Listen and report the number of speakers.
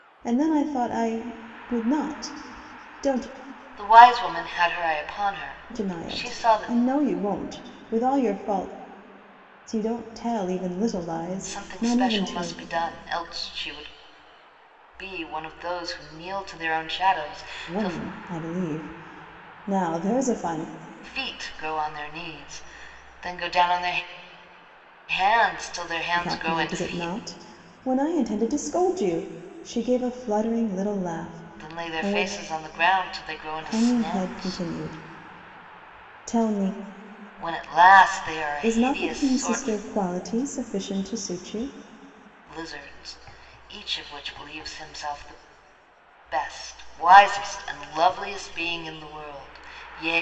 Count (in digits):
2